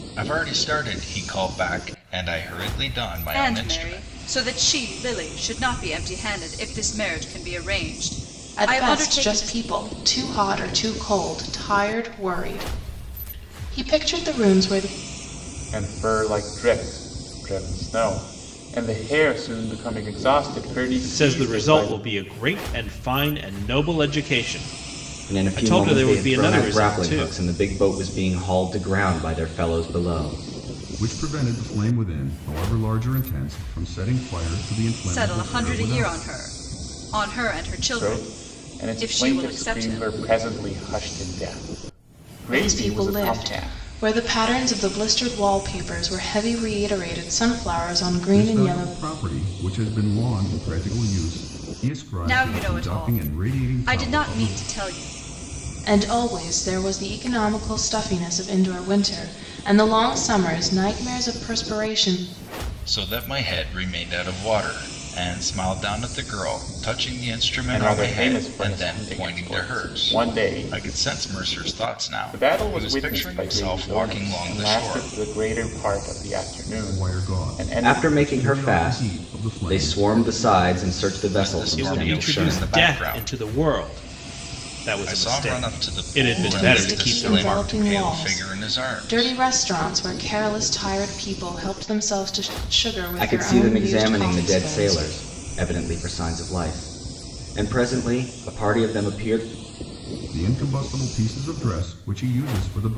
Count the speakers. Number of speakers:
seven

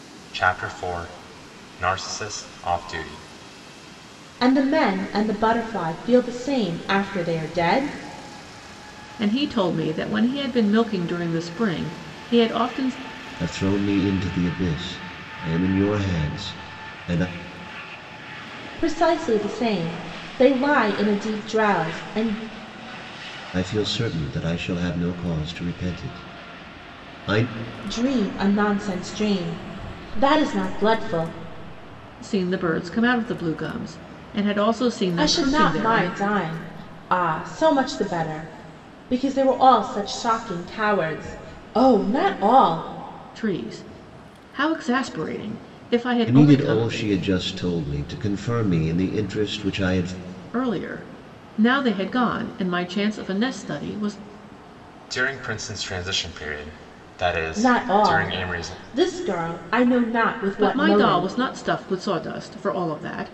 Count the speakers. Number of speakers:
four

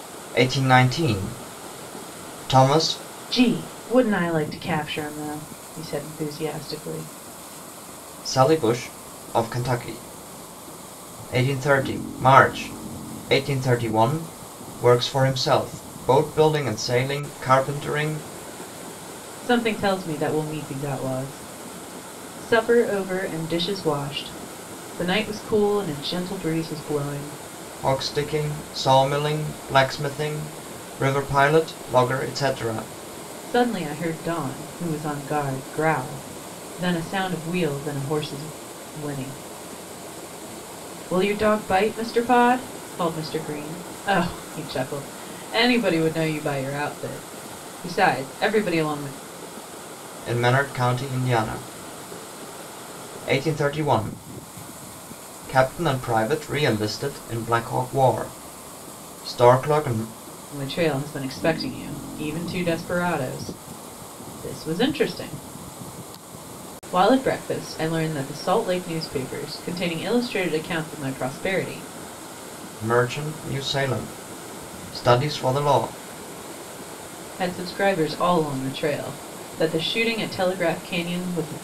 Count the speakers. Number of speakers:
two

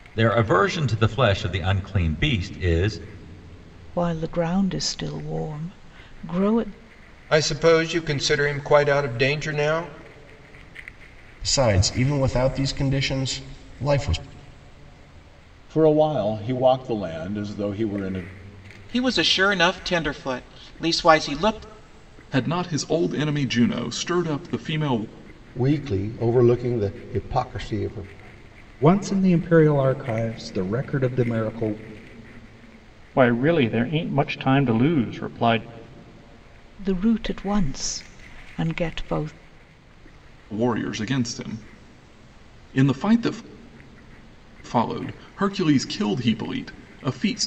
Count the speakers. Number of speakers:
ten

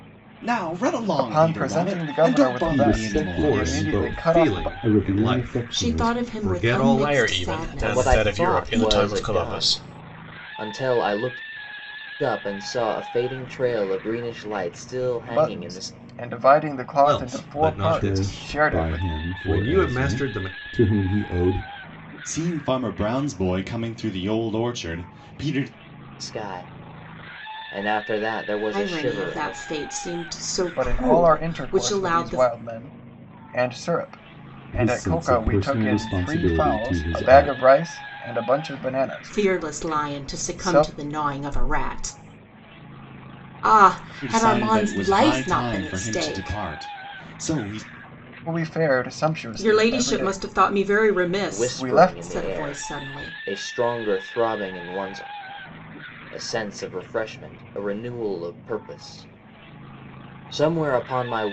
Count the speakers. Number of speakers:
seven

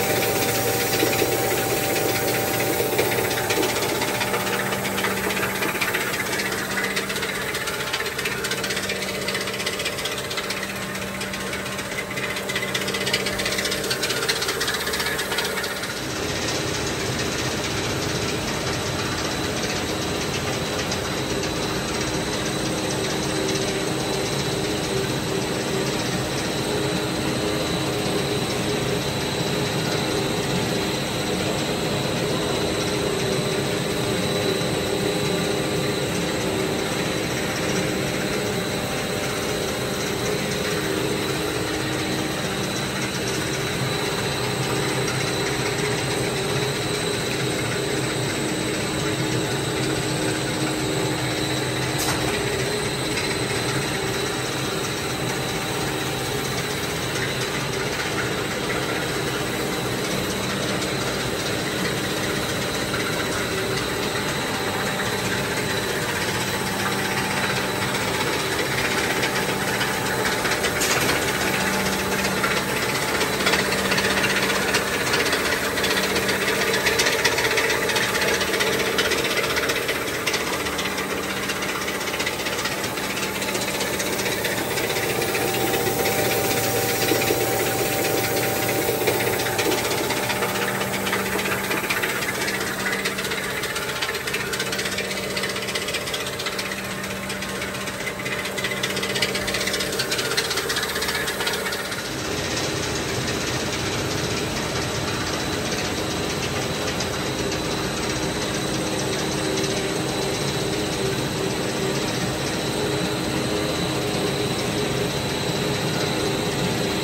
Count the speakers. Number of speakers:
zero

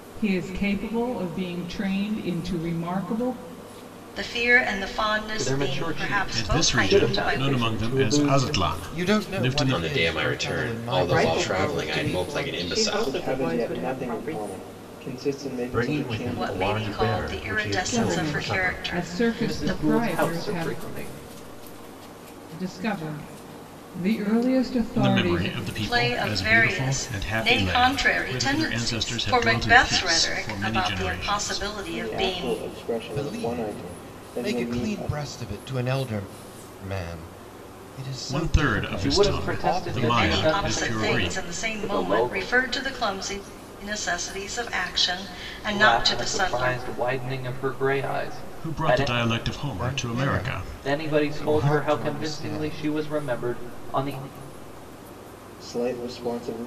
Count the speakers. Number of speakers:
nine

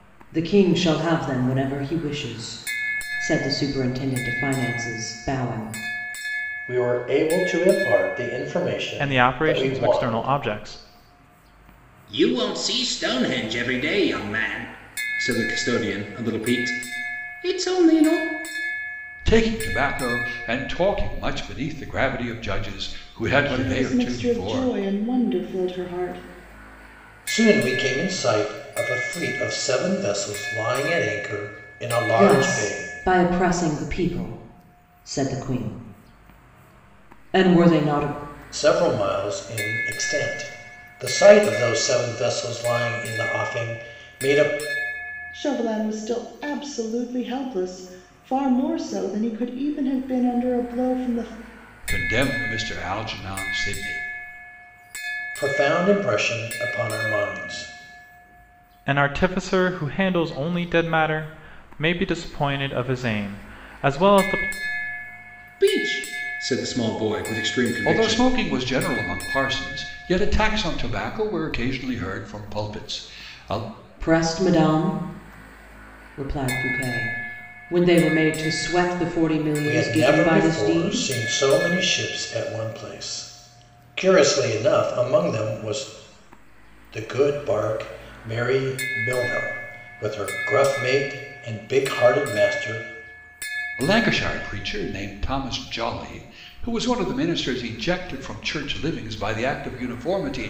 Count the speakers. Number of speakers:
six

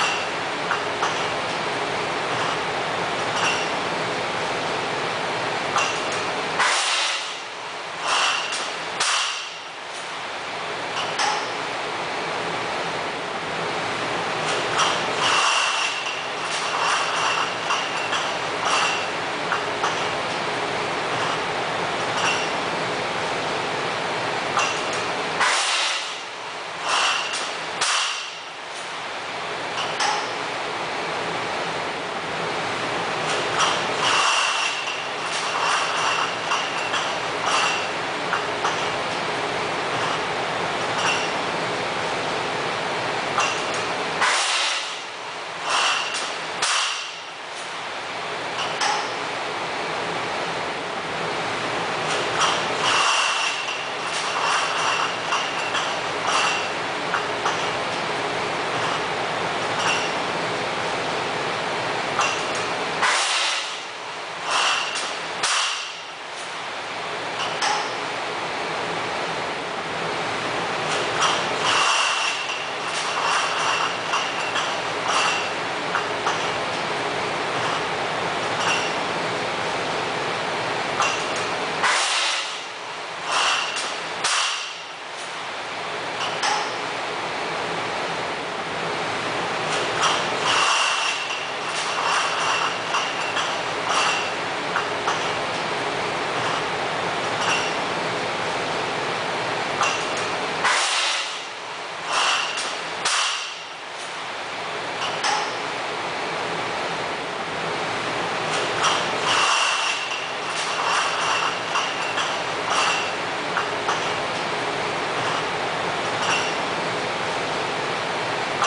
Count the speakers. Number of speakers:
zero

